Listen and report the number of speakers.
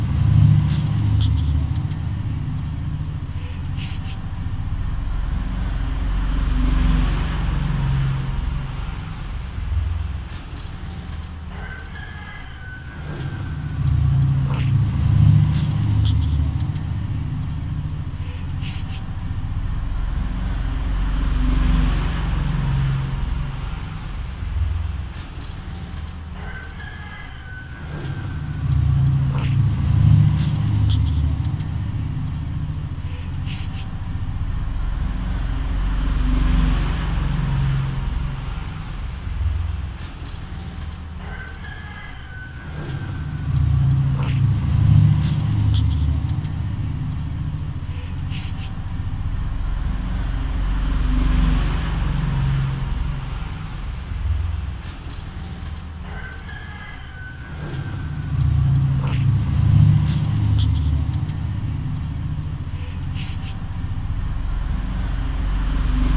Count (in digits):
0